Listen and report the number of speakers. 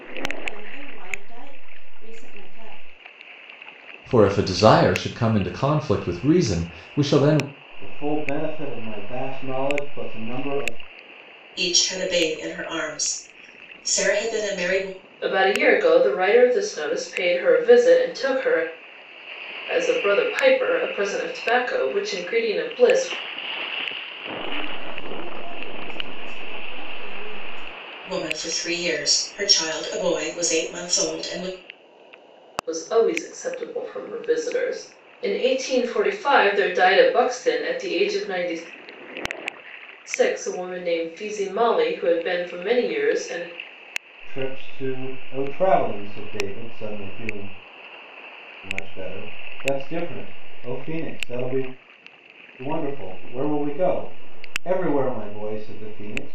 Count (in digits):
5